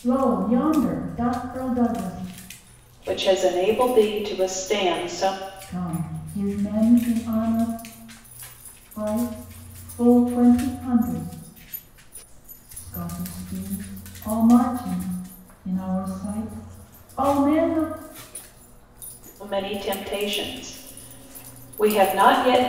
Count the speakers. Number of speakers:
2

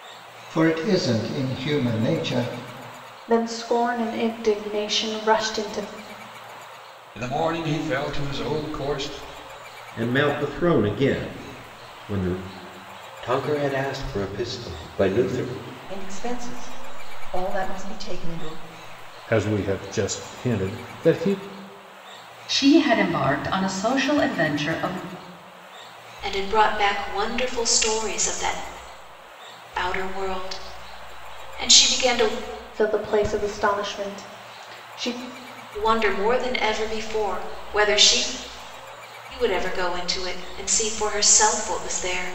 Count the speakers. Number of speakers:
9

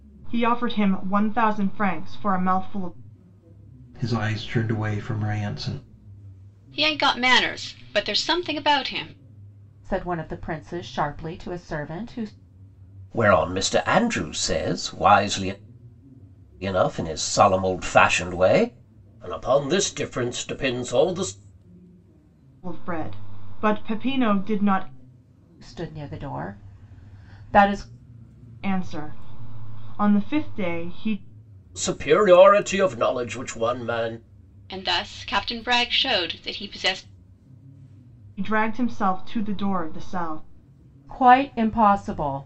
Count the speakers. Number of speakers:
5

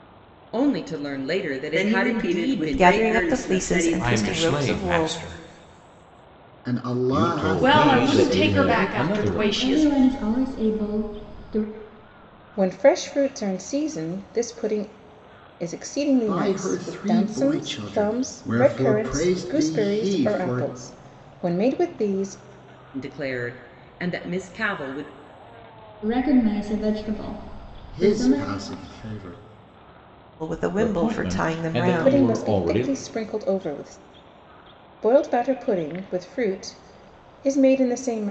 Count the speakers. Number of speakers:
9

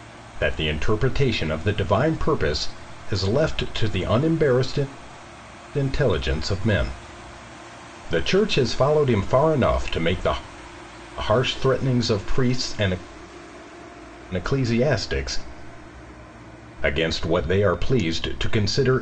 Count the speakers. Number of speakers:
1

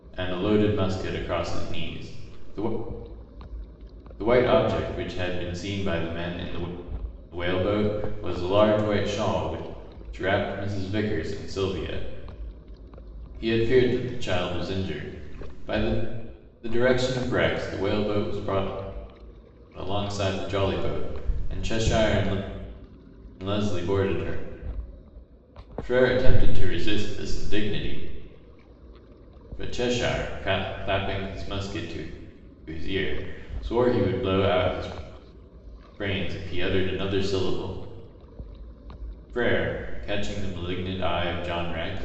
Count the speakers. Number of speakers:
1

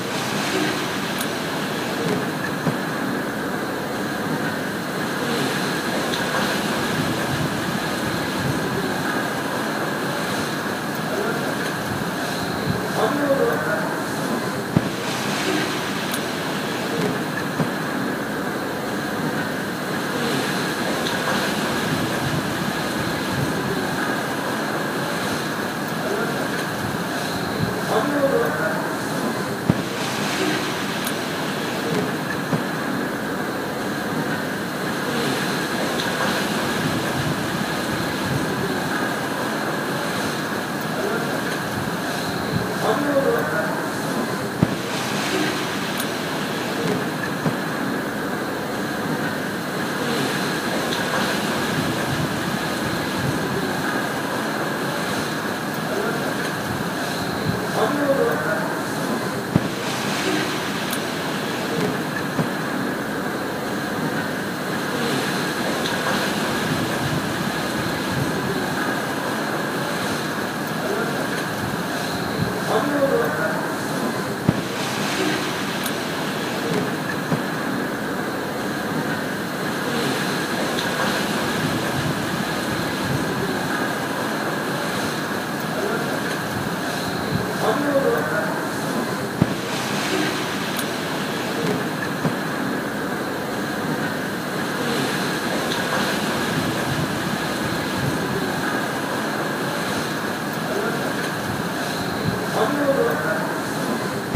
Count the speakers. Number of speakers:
0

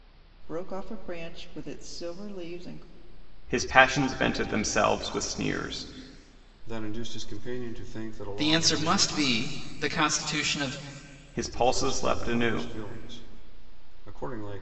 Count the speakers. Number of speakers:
4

